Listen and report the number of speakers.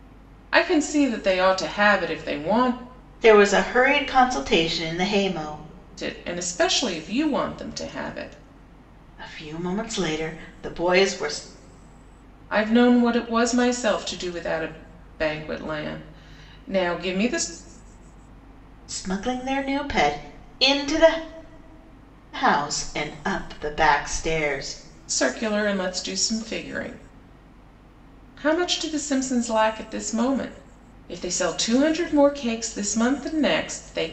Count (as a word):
two